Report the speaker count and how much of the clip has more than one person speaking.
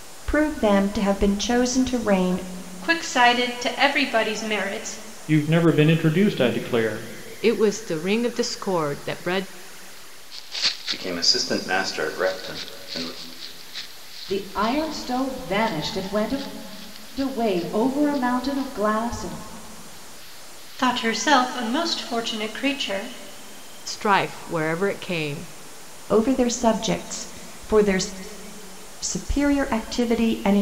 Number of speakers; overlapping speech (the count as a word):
six, no overlap